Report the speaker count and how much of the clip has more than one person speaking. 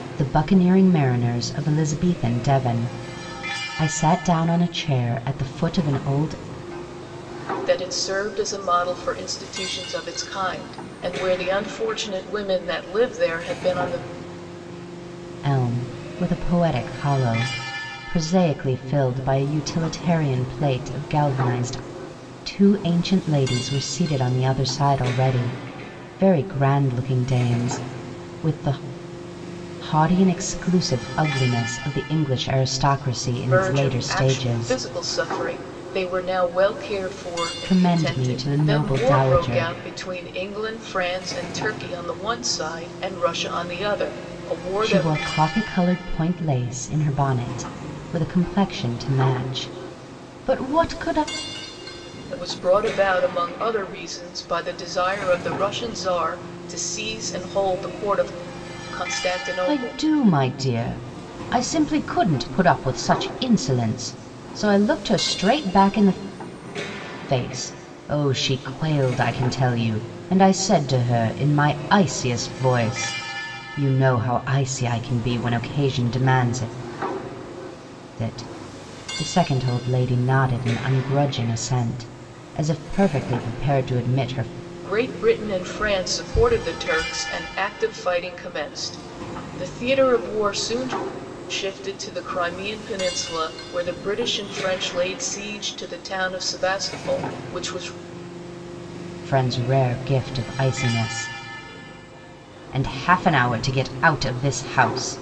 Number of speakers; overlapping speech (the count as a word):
two, about 4%